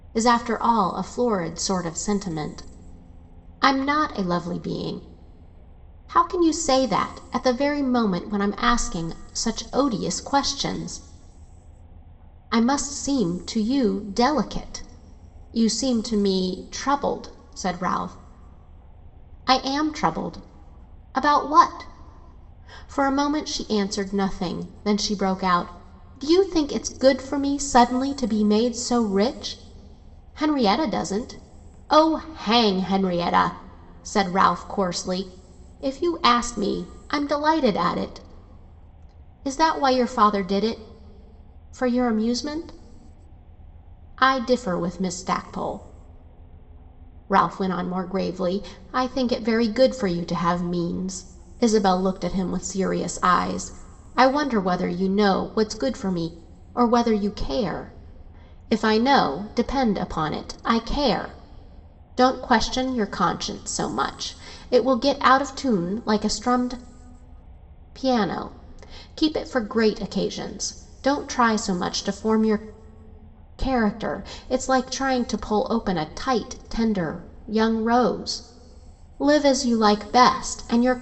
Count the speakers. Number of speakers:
1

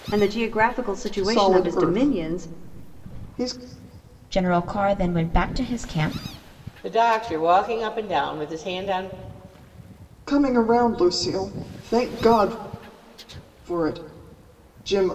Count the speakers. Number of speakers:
4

